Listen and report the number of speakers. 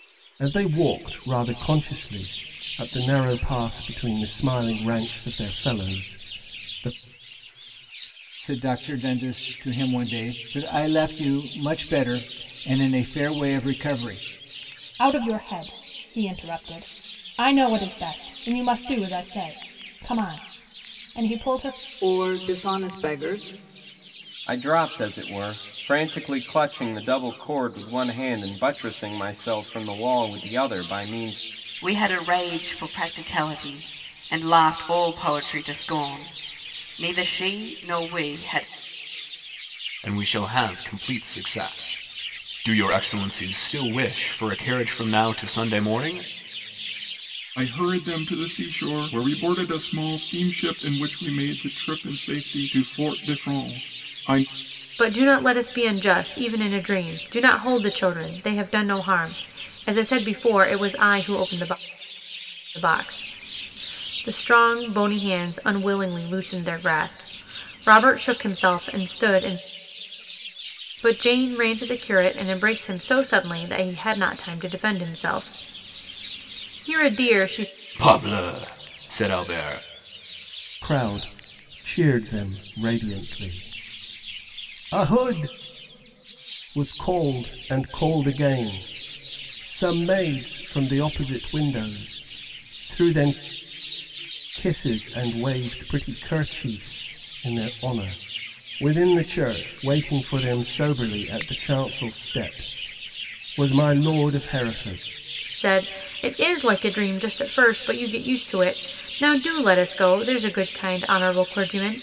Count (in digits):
9